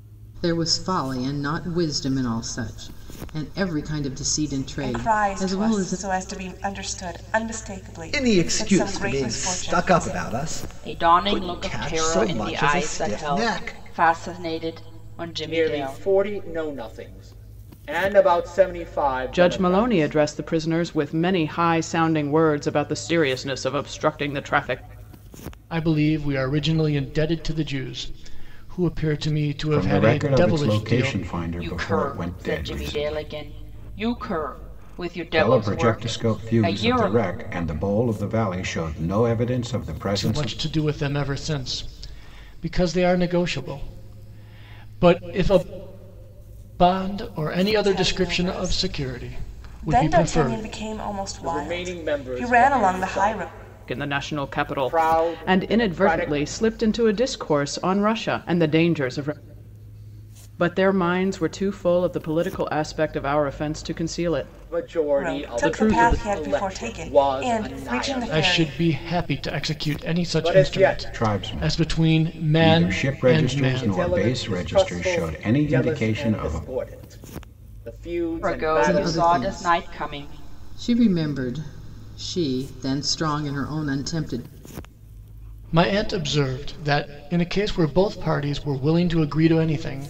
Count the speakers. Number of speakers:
8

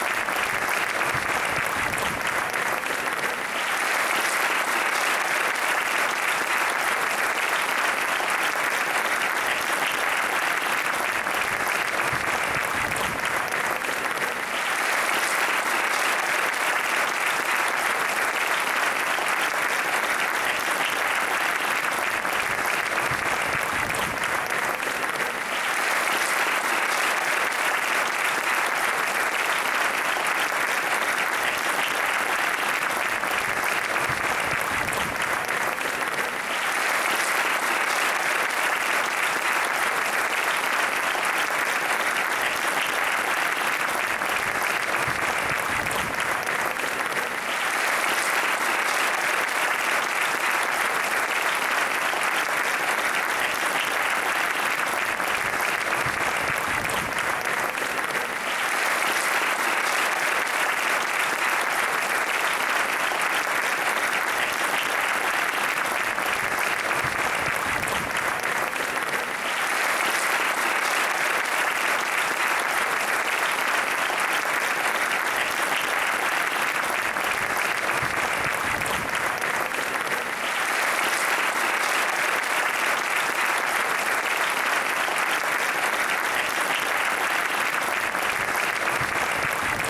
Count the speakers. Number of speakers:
0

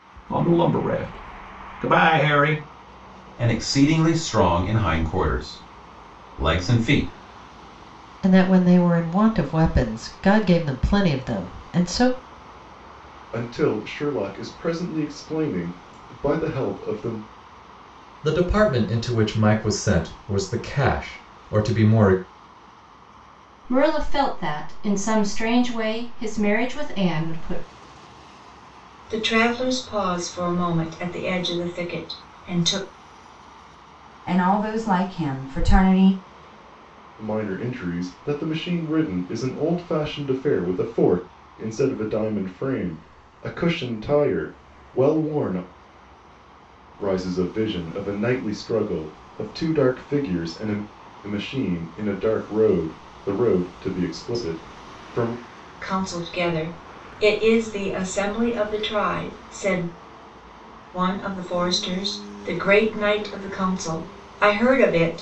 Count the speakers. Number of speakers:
8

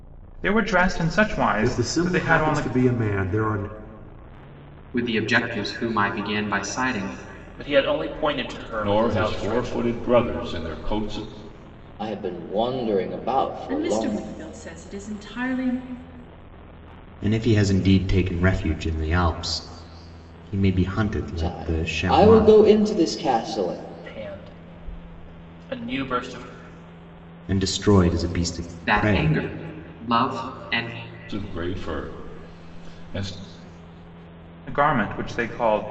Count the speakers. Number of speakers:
8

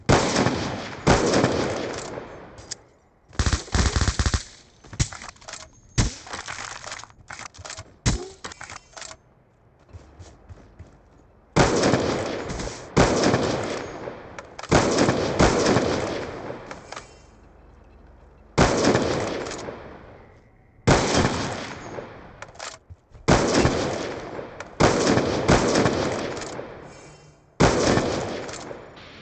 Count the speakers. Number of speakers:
0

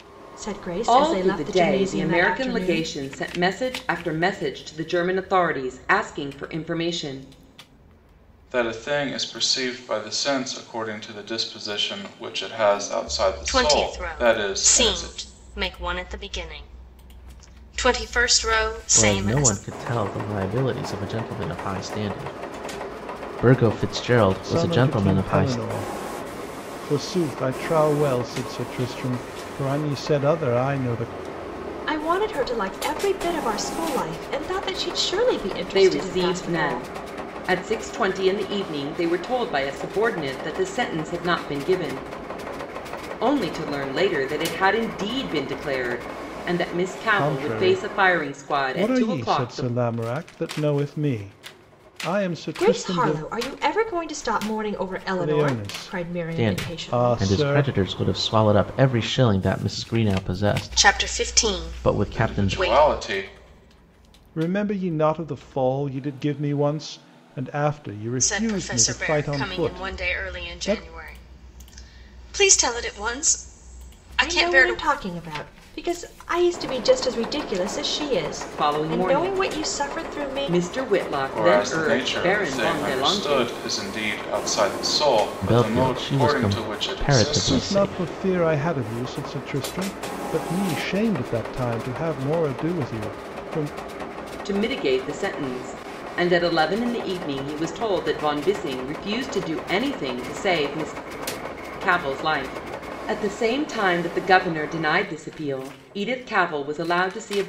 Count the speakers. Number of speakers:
6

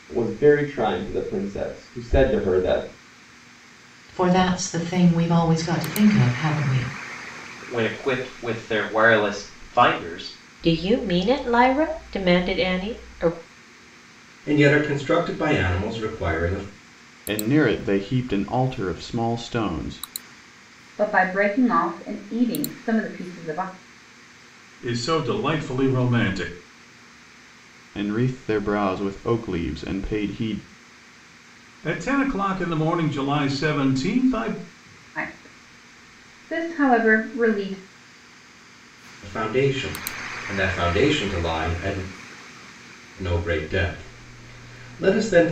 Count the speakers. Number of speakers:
8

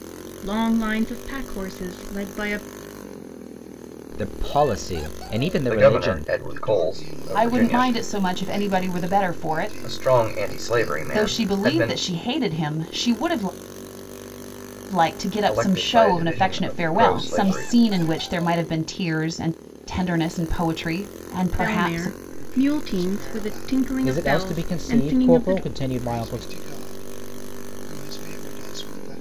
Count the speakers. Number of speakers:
5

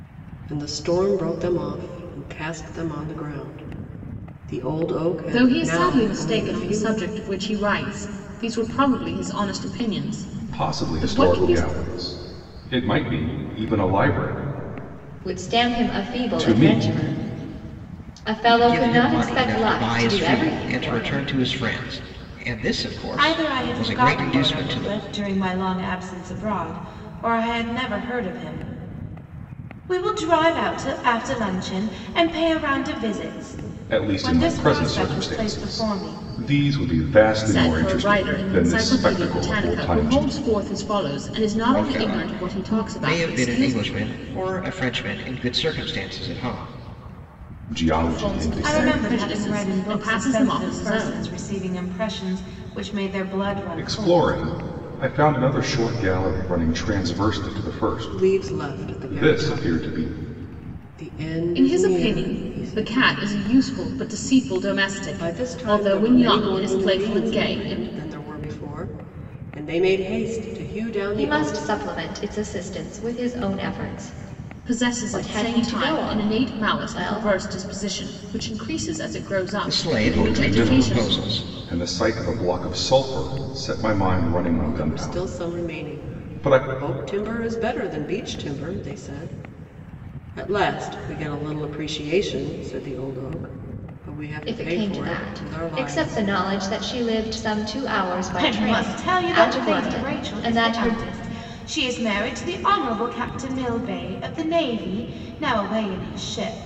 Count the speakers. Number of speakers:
6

